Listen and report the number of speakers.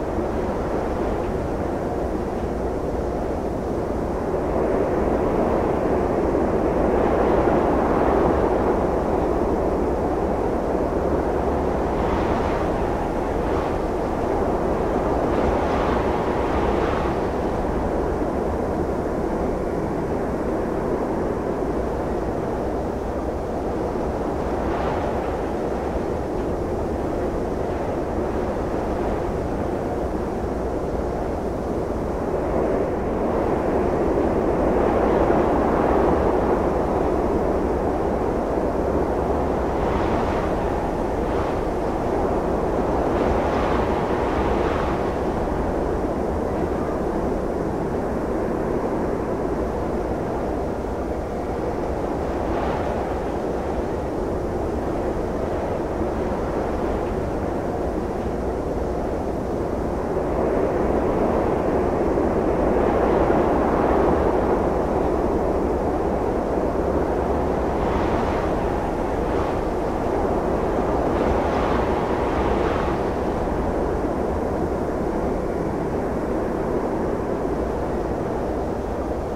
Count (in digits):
0